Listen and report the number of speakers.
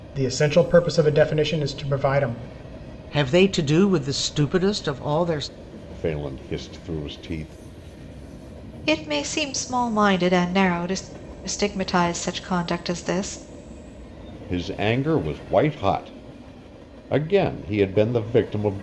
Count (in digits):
4